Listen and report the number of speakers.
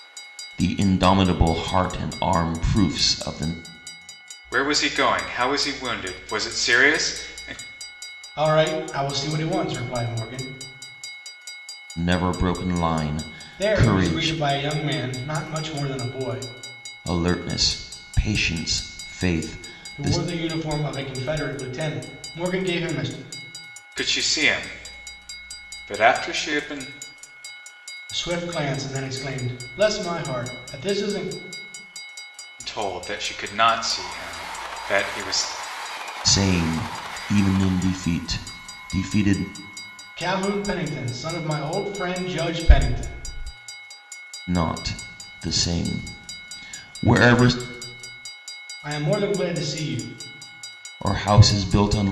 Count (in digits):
3